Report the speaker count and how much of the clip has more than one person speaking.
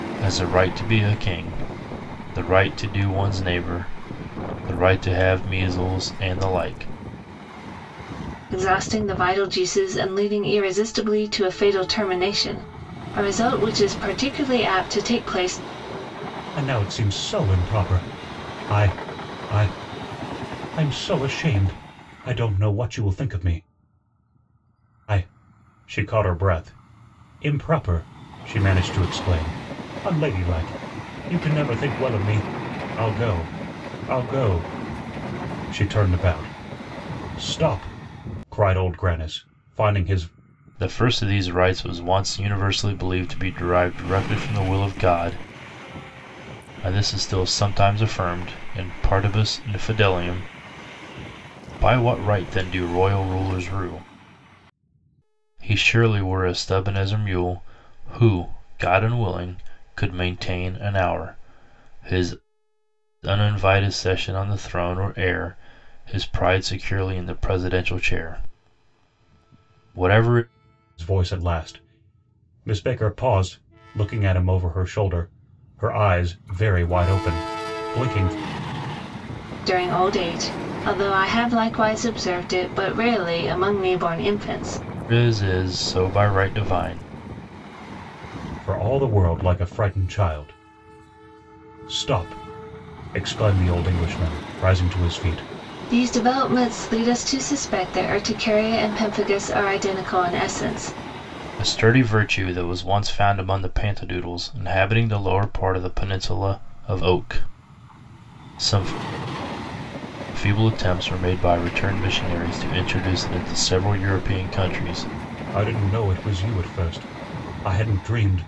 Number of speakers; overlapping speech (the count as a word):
three, no overlap